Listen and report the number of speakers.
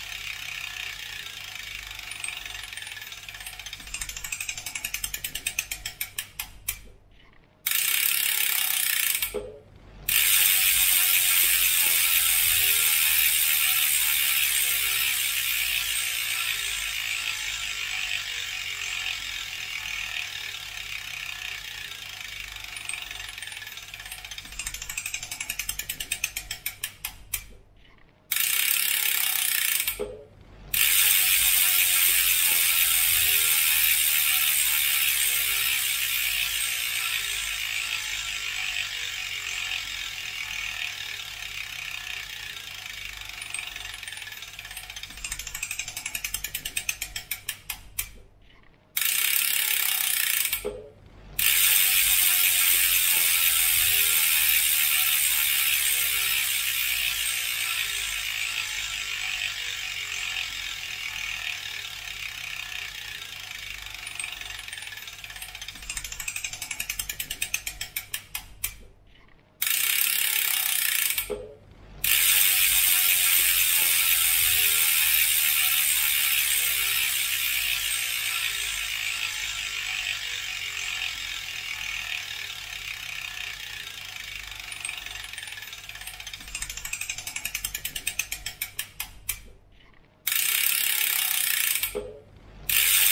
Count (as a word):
zero